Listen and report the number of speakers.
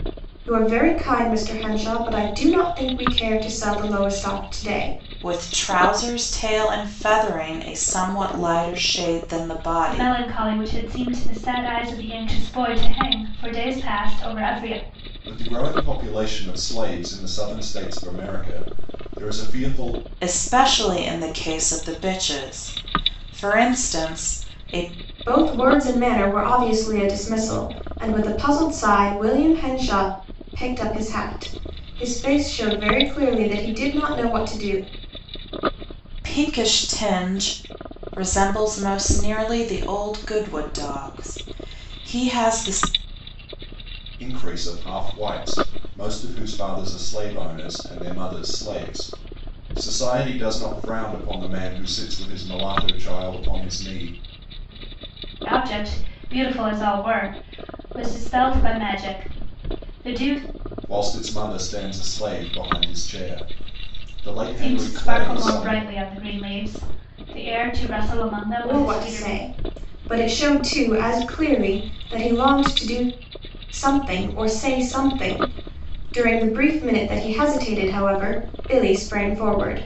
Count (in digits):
4